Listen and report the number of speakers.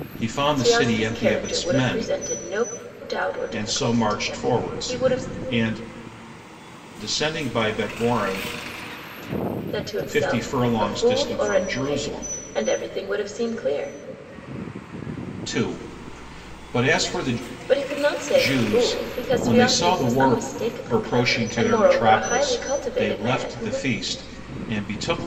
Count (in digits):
2